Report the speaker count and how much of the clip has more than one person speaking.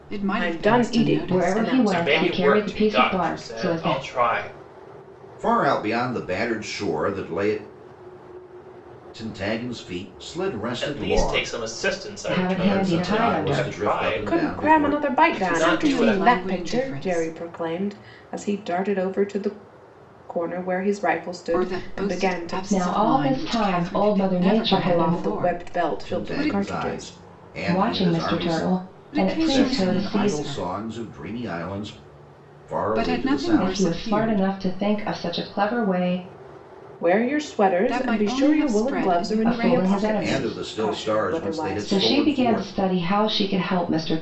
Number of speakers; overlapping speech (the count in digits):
5, about 55%